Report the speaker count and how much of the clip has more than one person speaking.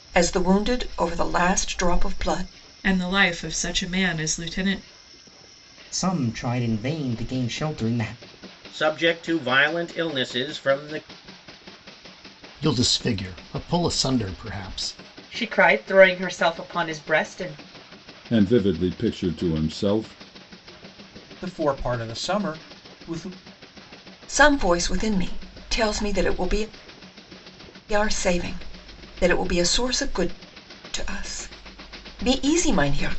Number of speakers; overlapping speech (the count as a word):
eight, no overlap